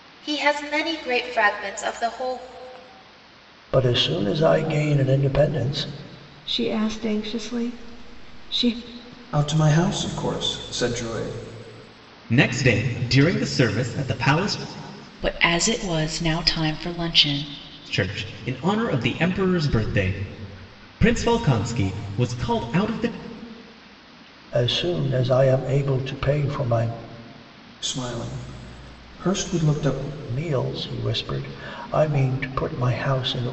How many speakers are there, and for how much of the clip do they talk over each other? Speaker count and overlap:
6, no overlap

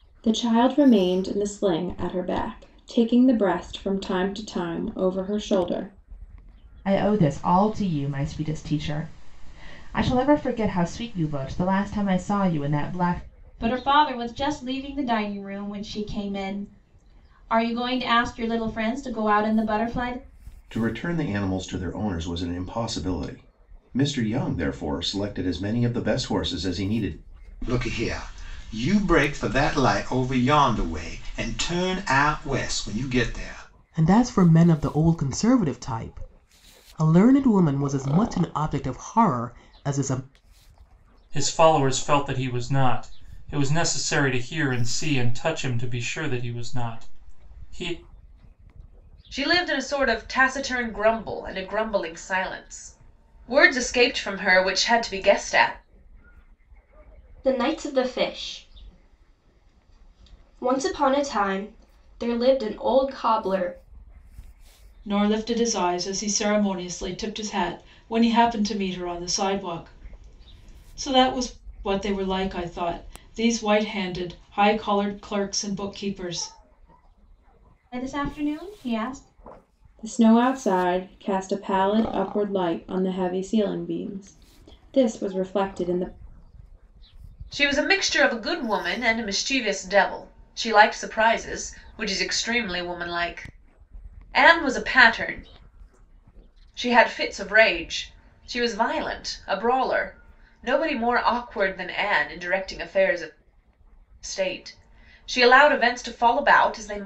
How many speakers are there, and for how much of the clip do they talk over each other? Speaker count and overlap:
10, no overlap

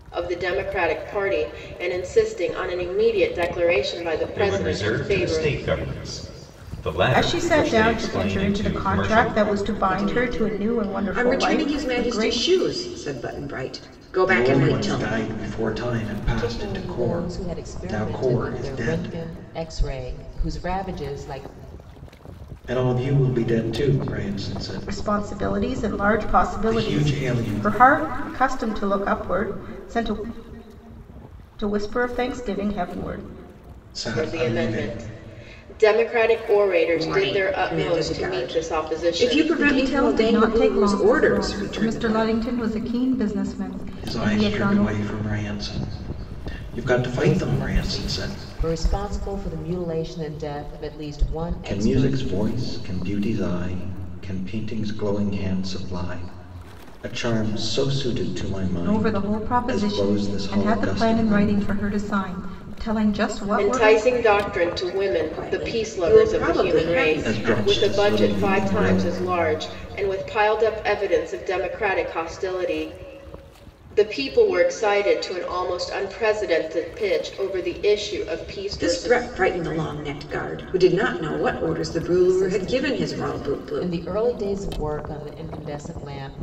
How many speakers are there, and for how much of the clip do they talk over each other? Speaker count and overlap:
6, about 36%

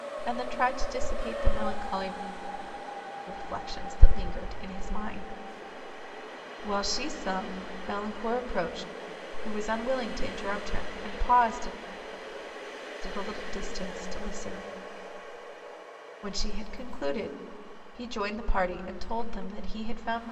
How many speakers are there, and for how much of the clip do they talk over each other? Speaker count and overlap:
1, no overlap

